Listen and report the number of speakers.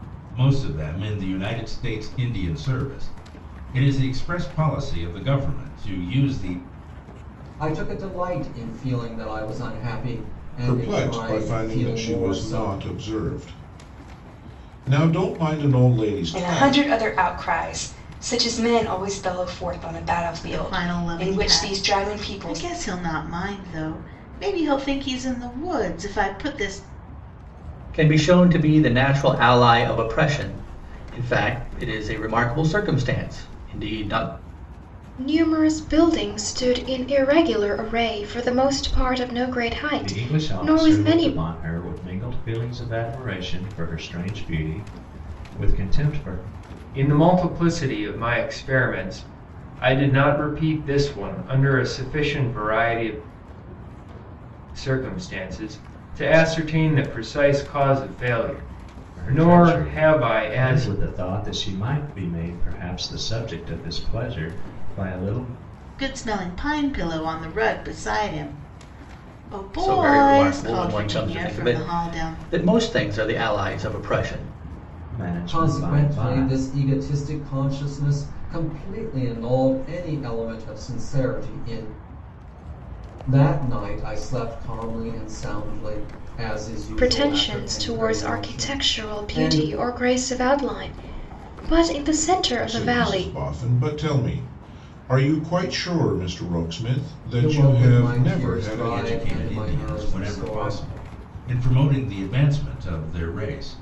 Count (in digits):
9